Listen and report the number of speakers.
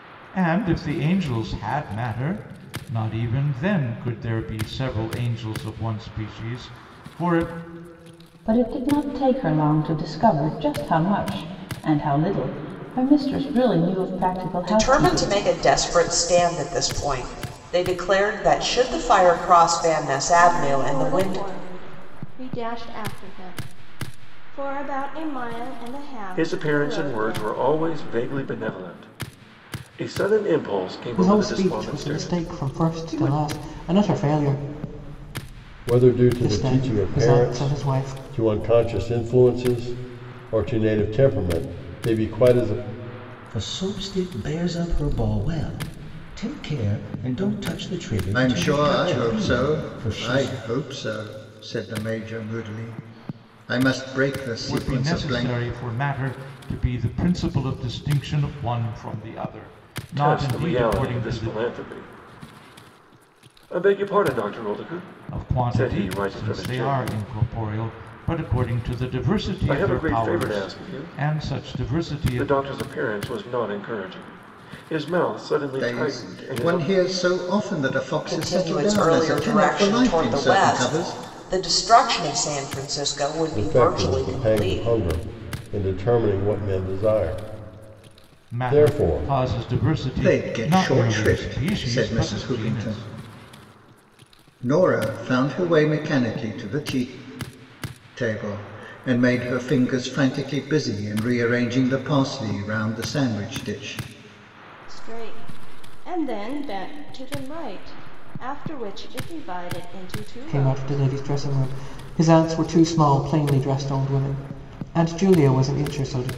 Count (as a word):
nine